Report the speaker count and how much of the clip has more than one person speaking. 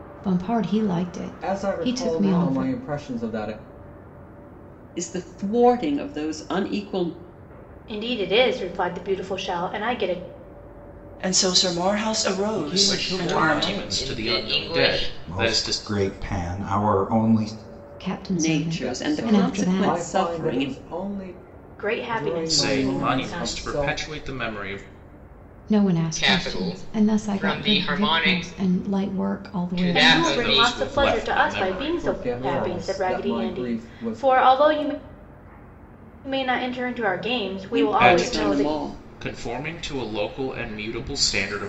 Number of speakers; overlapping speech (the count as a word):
nine, about 41%